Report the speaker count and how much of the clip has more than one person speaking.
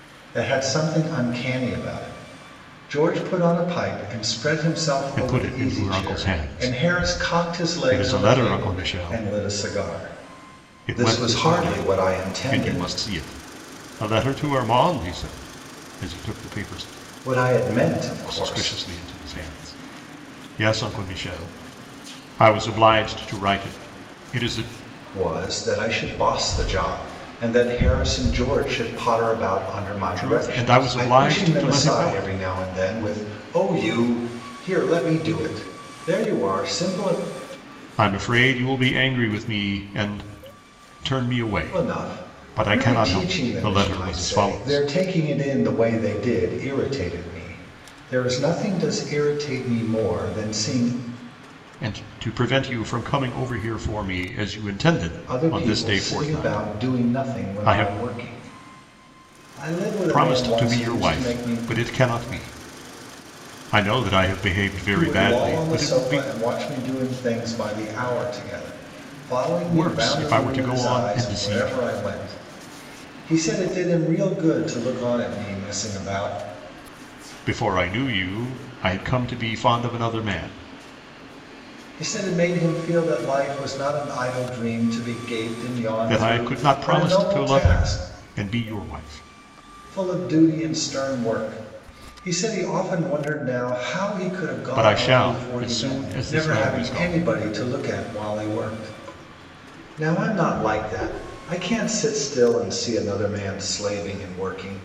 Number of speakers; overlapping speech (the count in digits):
2, about 23%